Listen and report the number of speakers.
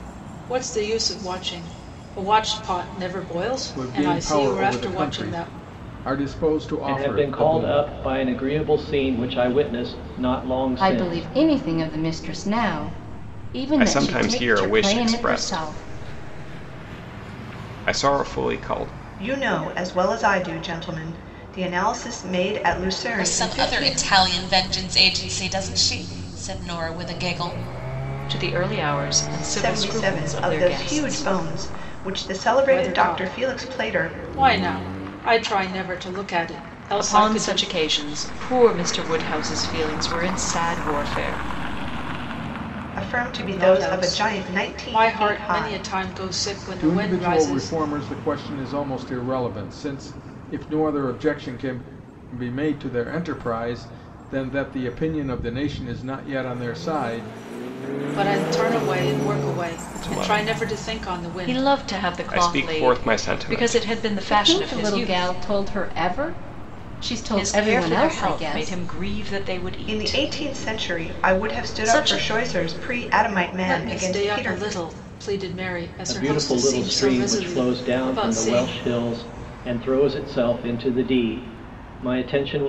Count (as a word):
eight